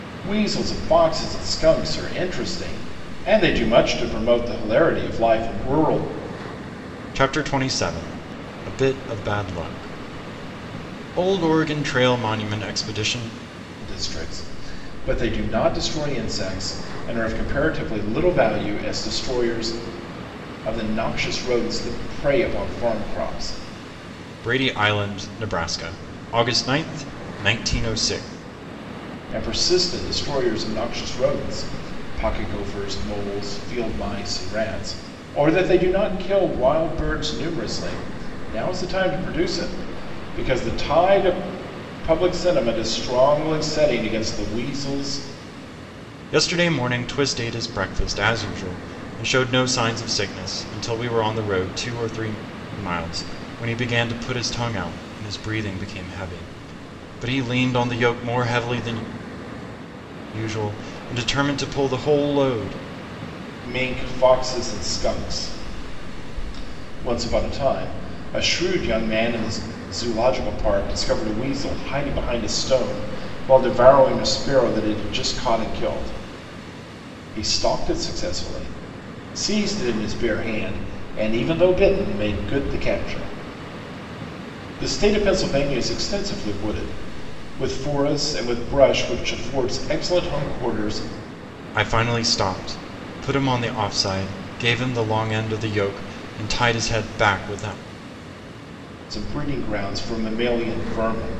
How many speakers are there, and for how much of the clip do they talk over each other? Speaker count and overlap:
two, no overlap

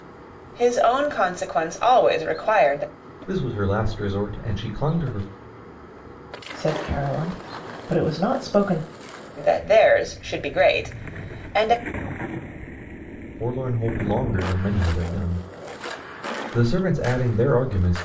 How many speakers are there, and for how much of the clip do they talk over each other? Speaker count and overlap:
three, no overlap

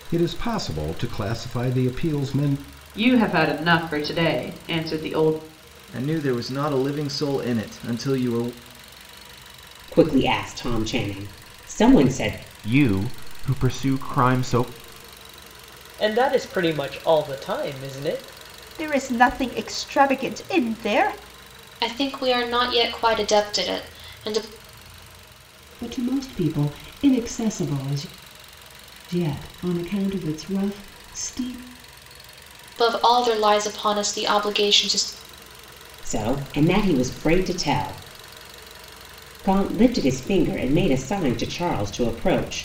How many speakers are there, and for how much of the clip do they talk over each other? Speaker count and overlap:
nine, no overlap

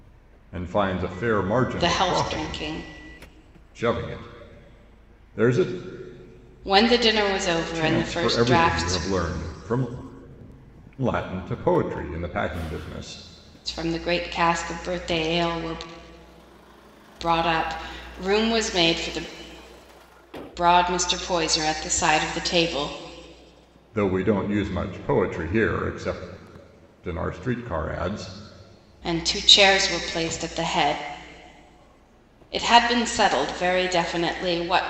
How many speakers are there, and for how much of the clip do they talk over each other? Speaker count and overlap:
two, about 6%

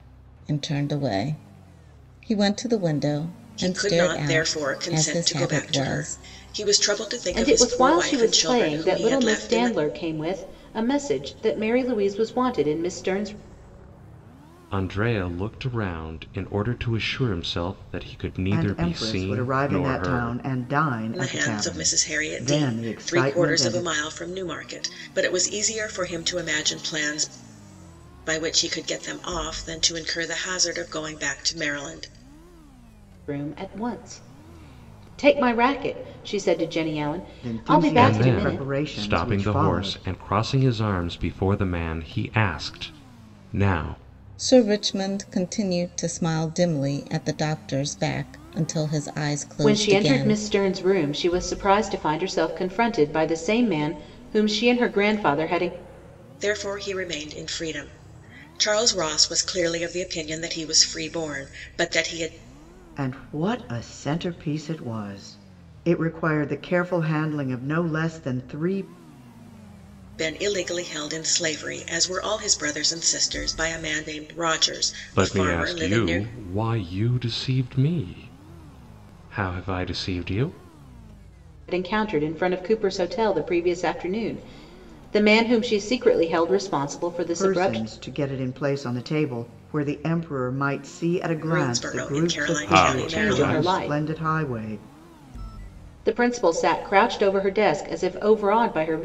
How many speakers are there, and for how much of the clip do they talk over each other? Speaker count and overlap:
five, about 18%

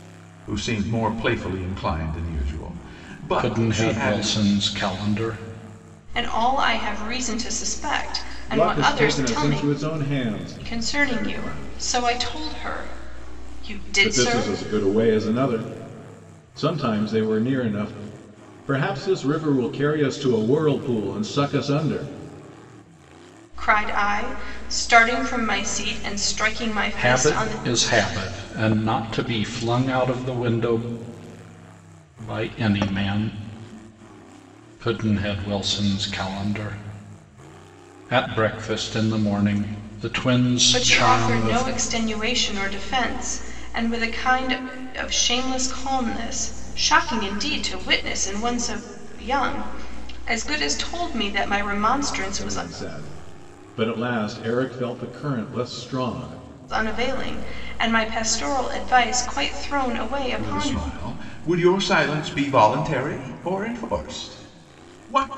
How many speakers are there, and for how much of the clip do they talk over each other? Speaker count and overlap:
four, about 10%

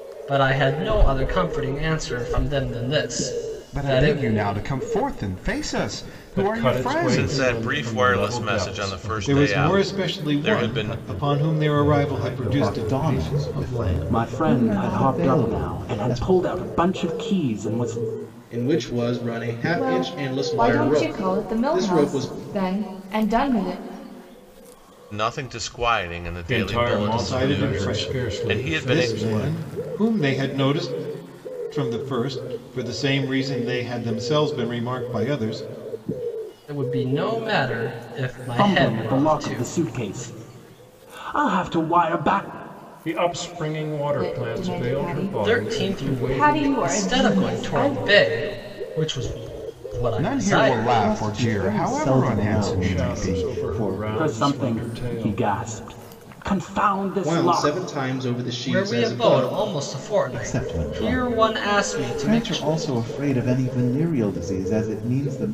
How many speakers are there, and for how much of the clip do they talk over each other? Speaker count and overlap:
ten, about 48%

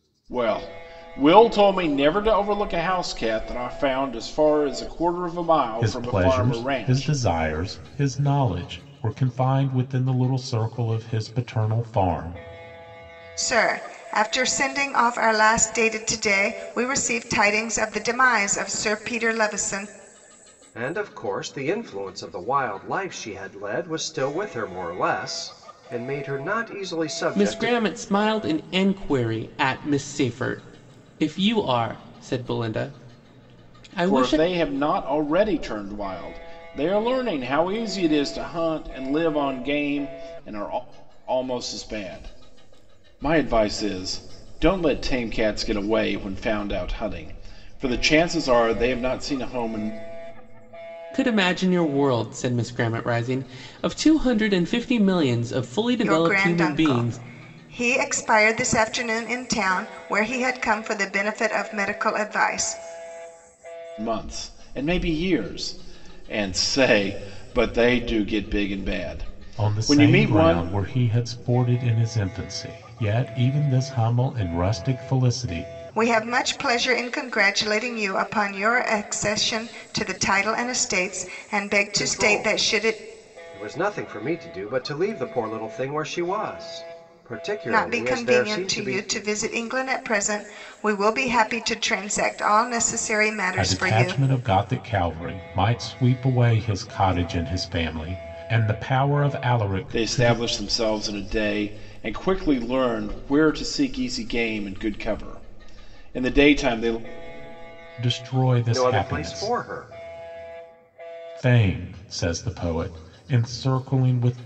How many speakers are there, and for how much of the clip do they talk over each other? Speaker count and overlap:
five, about 8%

